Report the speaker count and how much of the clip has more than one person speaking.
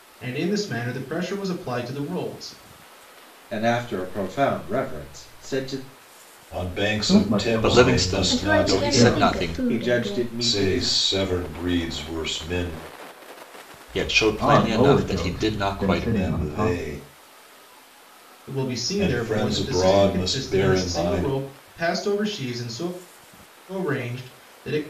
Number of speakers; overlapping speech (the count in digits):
6, about 35%